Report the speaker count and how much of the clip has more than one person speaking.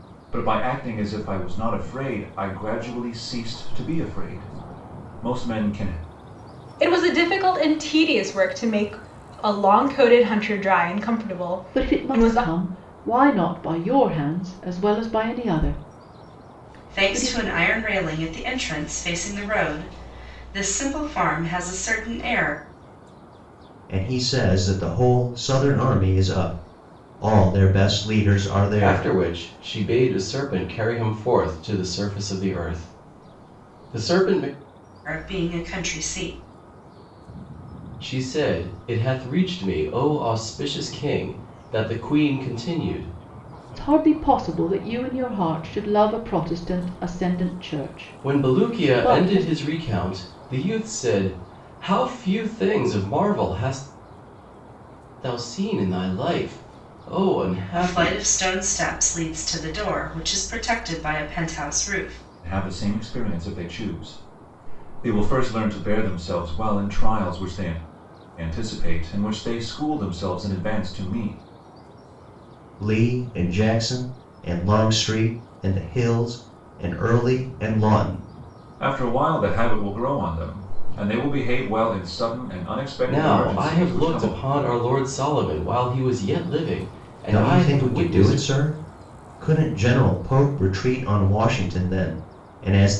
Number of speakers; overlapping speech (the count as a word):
six, about 6%